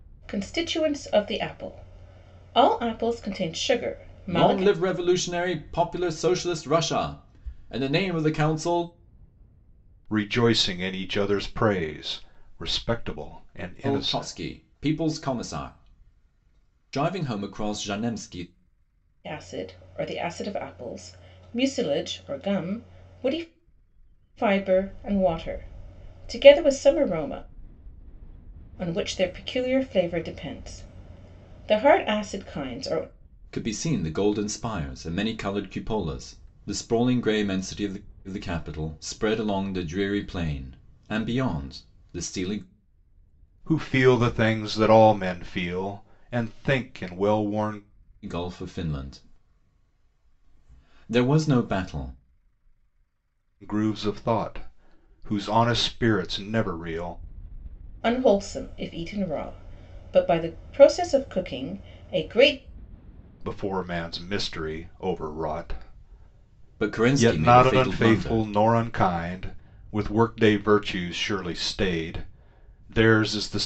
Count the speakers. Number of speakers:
three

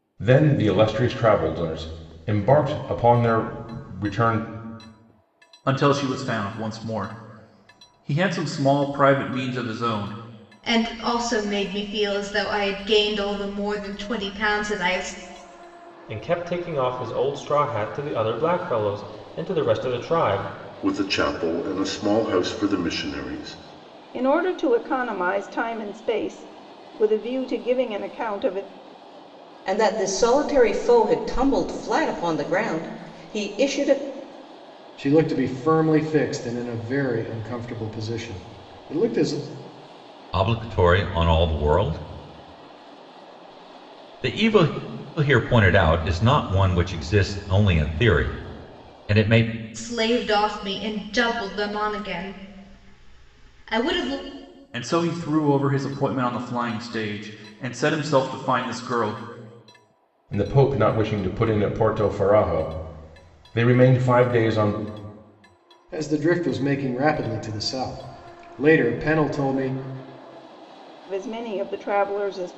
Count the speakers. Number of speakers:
nine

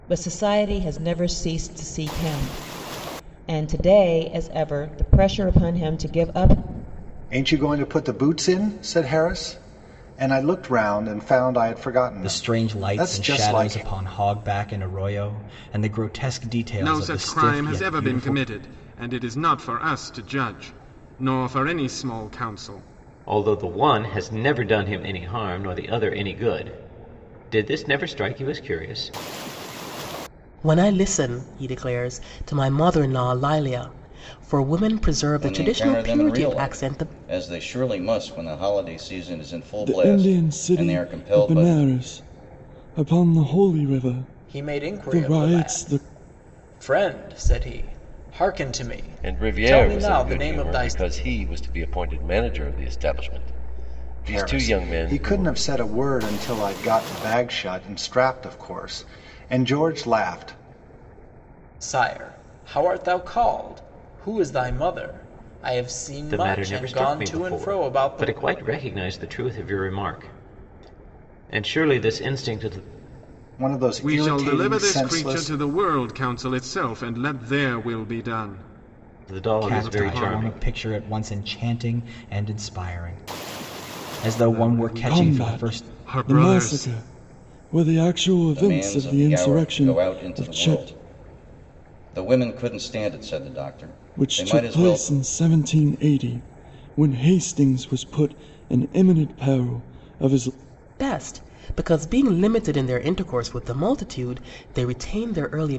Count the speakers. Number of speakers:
ten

